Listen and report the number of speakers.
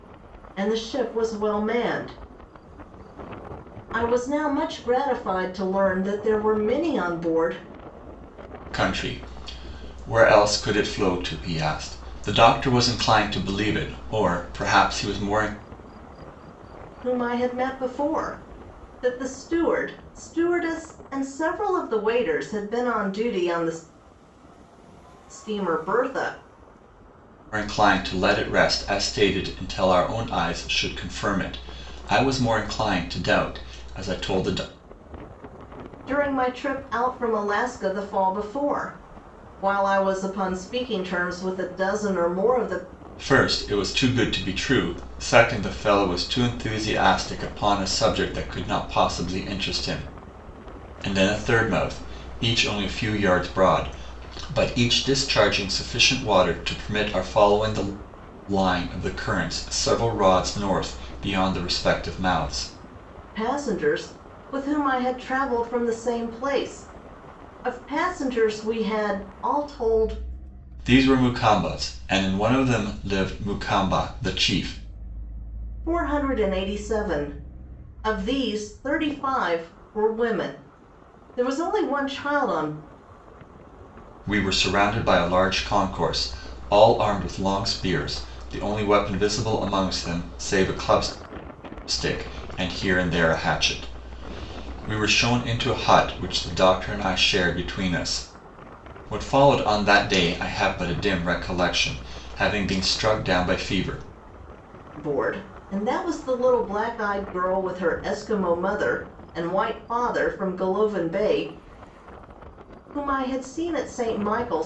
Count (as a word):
two